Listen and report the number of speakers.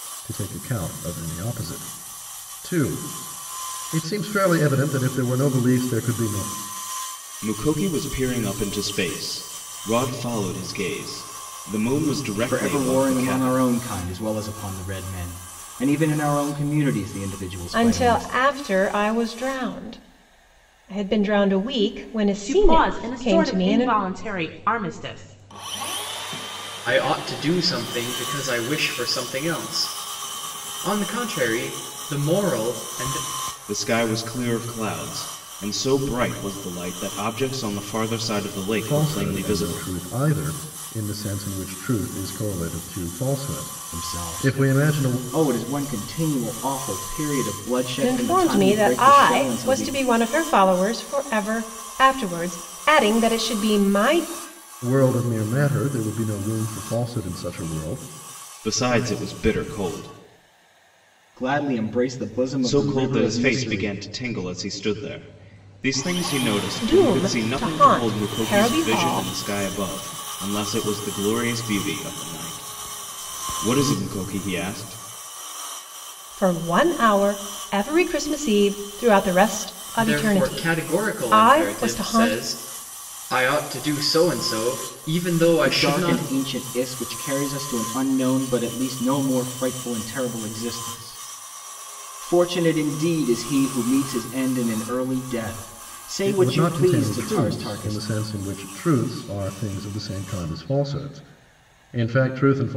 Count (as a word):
six